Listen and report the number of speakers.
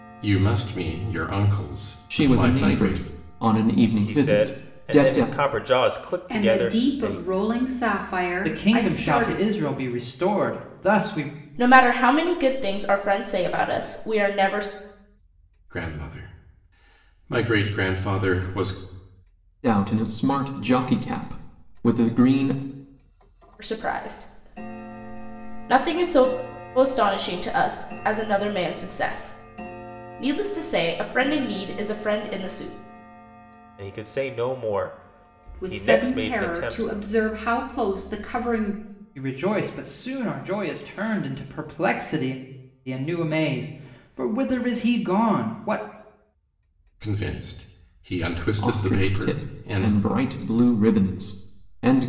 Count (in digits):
6